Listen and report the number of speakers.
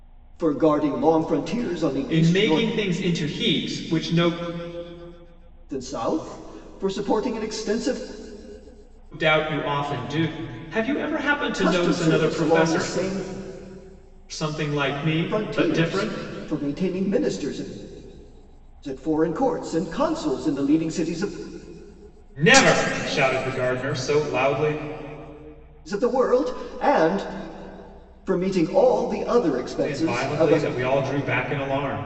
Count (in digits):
2